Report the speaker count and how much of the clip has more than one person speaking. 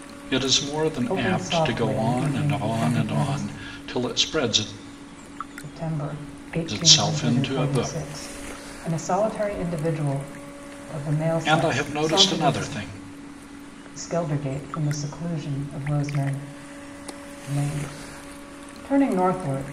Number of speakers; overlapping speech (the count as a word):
two, about 26%